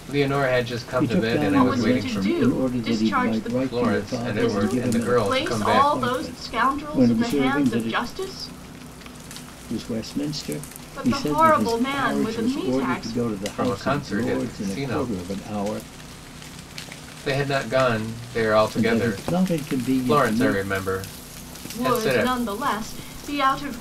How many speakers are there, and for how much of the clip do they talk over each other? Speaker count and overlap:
three, about 54%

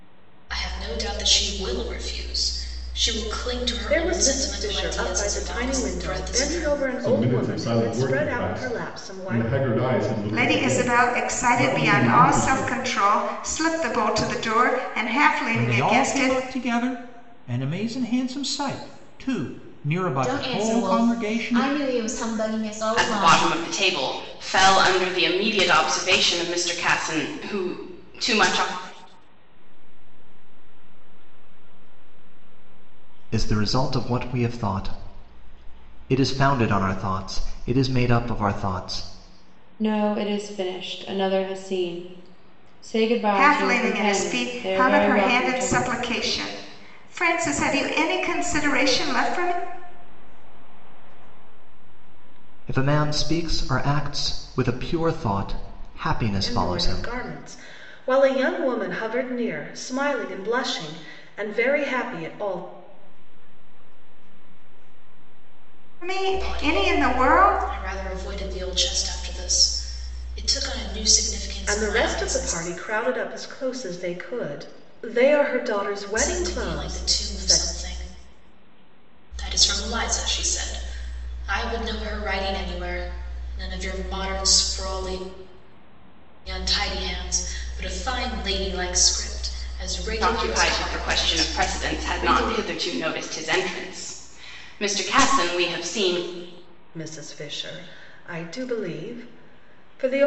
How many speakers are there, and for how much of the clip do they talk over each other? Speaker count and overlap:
ten, about 25%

